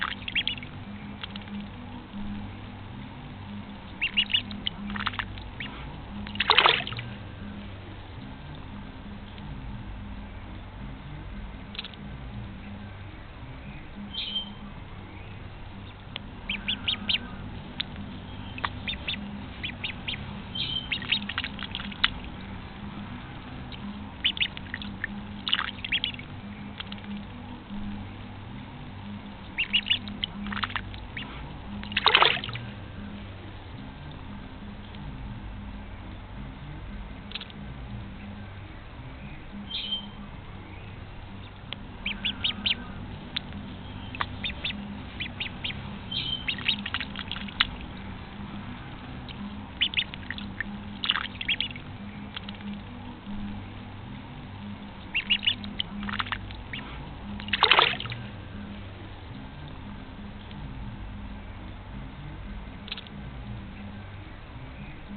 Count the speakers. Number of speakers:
zero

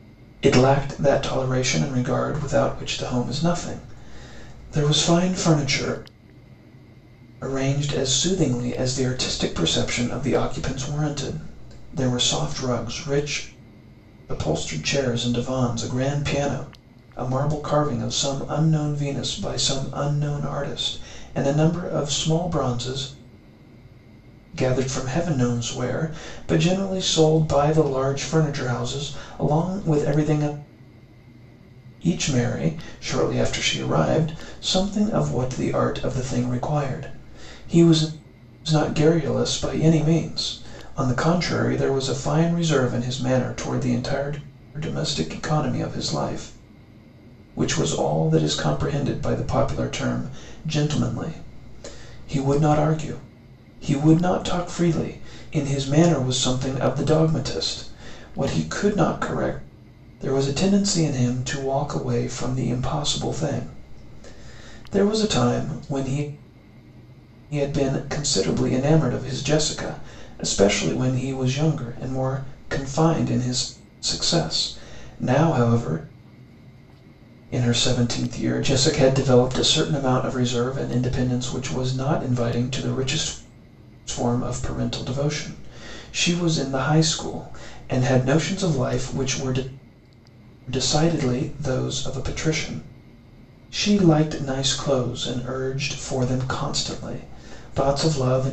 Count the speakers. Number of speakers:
one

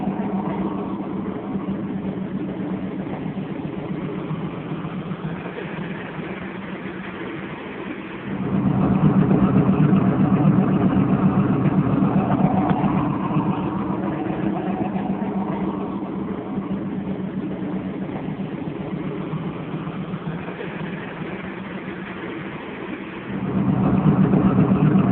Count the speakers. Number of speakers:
zero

